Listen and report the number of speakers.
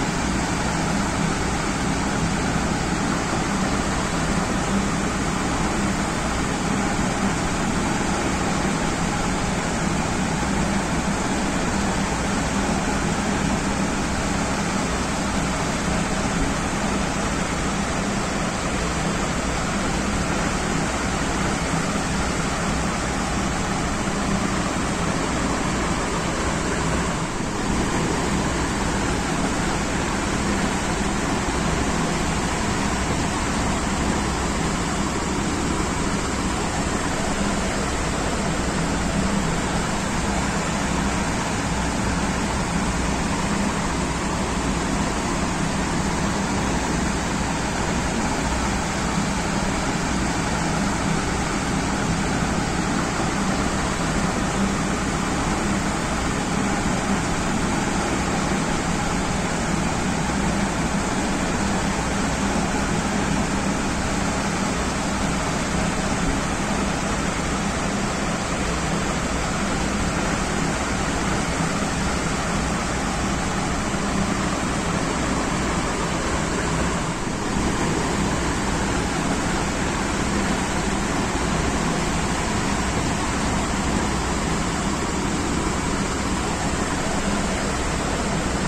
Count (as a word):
zero